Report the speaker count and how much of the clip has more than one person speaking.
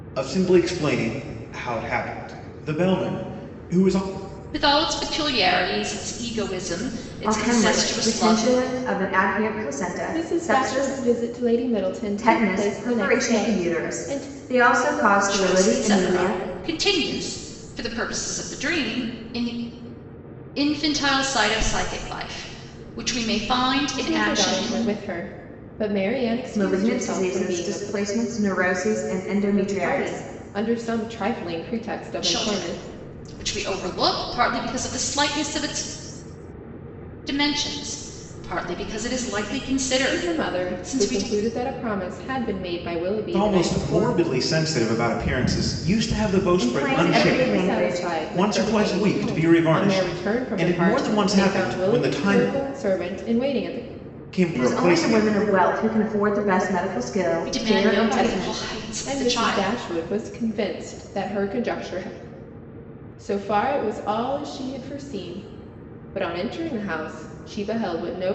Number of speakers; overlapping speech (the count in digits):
4, about 29%